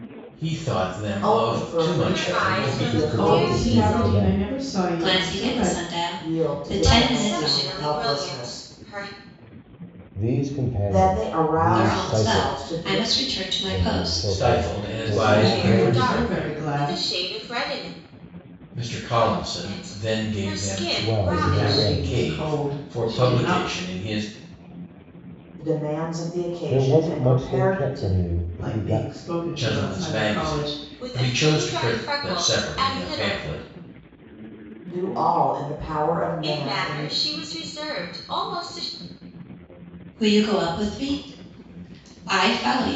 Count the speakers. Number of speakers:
six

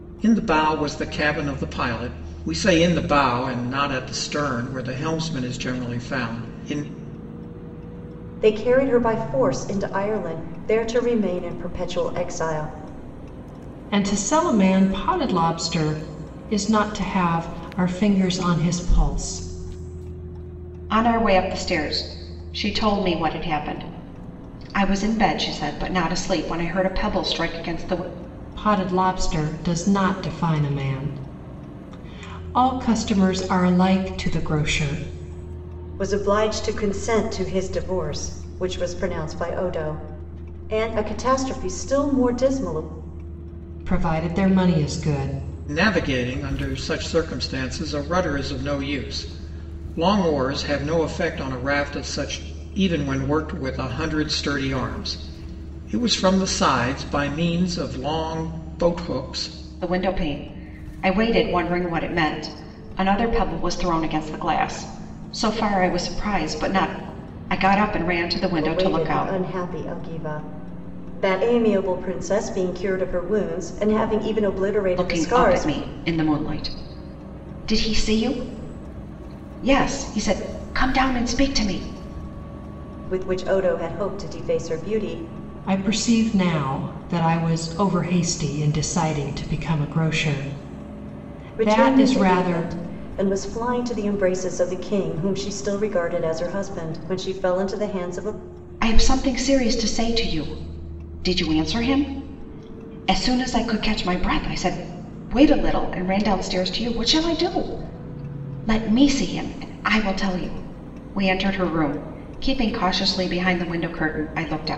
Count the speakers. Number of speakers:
four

